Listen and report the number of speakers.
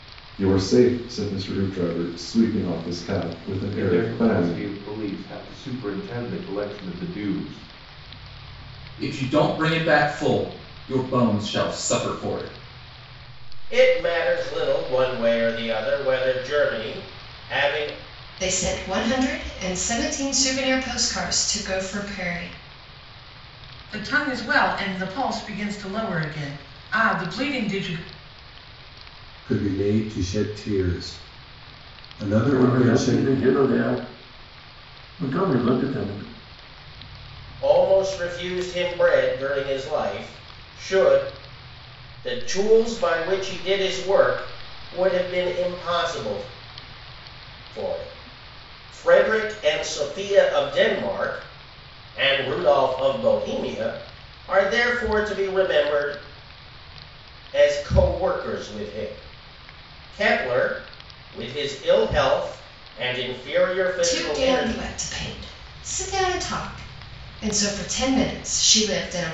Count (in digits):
8